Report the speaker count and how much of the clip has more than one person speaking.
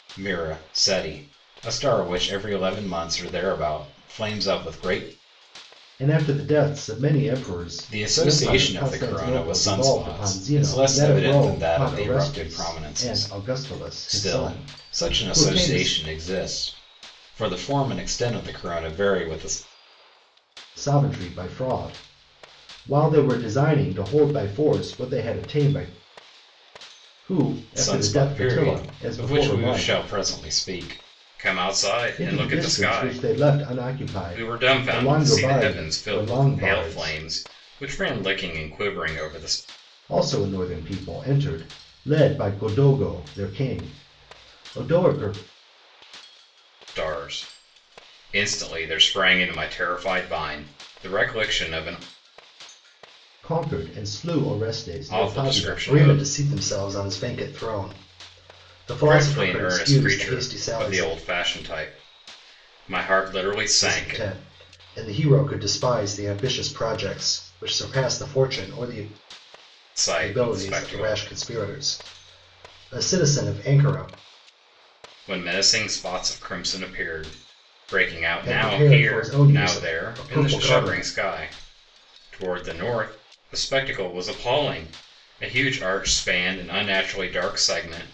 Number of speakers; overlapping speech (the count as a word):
two, about 24%